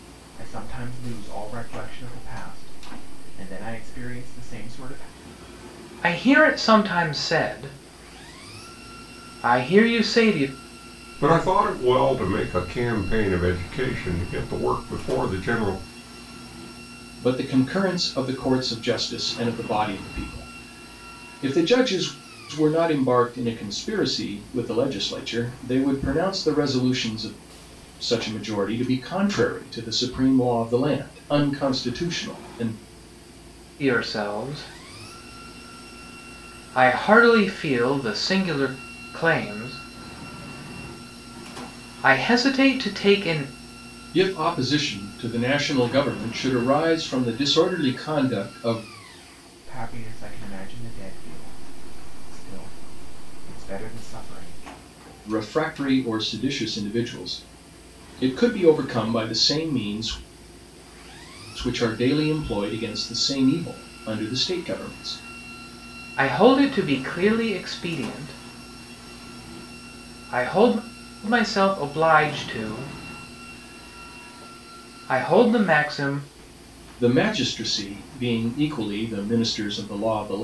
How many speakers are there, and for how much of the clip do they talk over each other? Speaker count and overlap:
4, no overlap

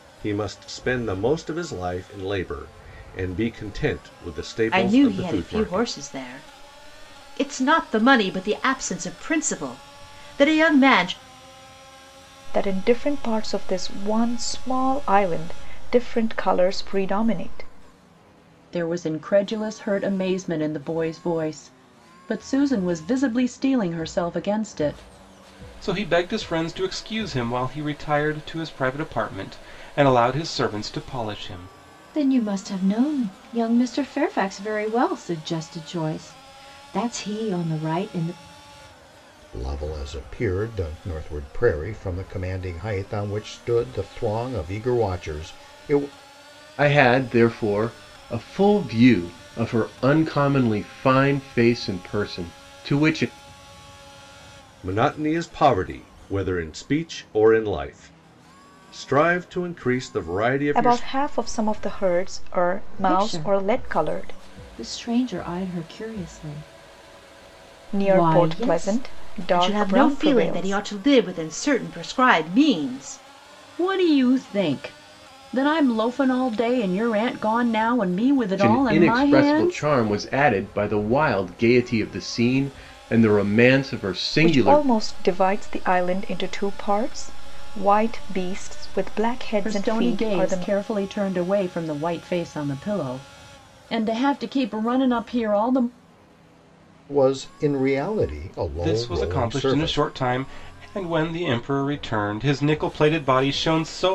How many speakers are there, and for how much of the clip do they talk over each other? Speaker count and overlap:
8, about 9%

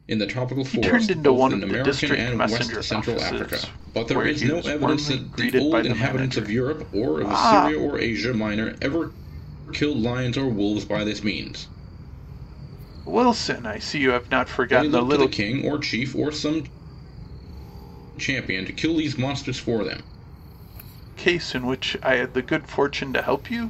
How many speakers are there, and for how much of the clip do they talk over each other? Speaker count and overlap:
2, about 33%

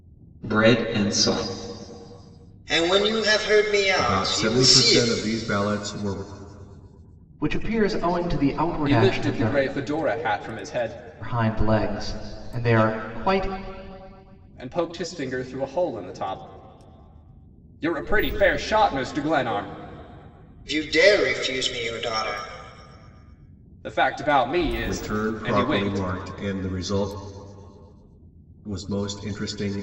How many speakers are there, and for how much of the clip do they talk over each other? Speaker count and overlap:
5, about 11%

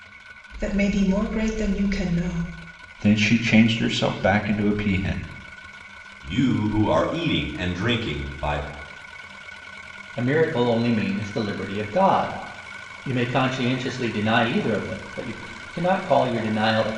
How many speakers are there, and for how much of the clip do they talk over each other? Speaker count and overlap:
4, no overlap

